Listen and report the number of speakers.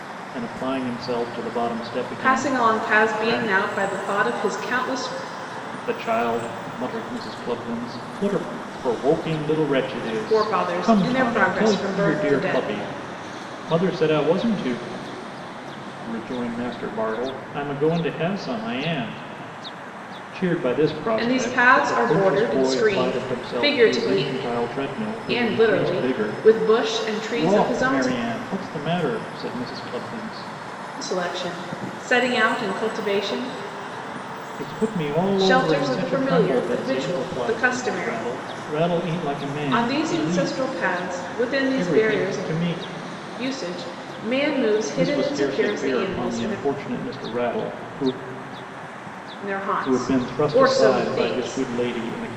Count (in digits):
2